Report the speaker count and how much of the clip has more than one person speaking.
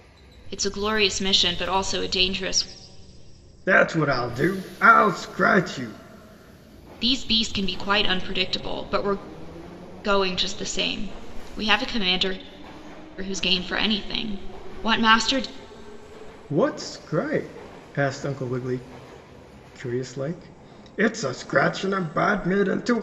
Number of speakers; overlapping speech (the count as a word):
two, no overlap